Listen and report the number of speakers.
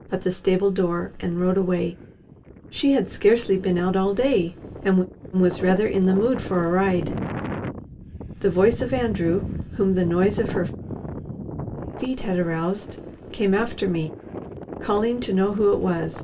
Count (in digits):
1